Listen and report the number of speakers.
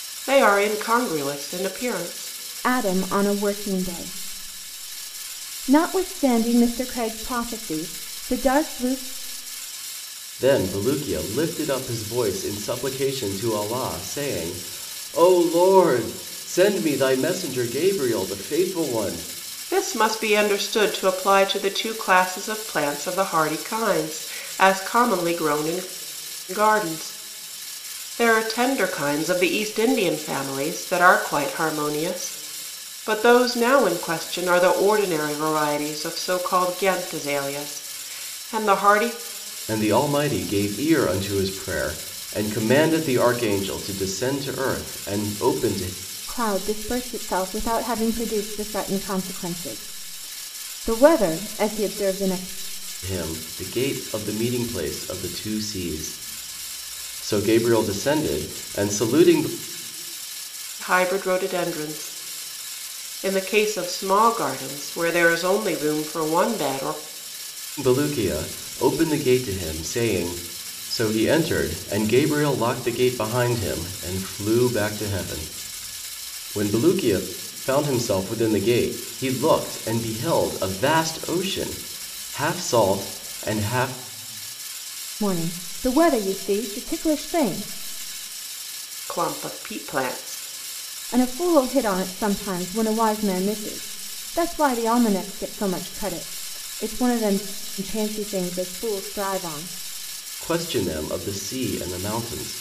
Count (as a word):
three